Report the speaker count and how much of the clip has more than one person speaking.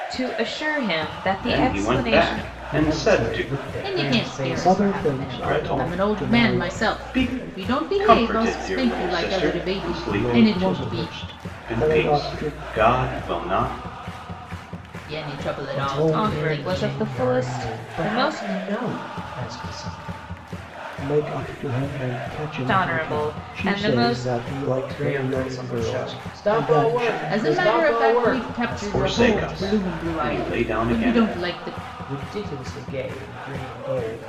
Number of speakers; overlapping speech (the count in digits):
5, about 59%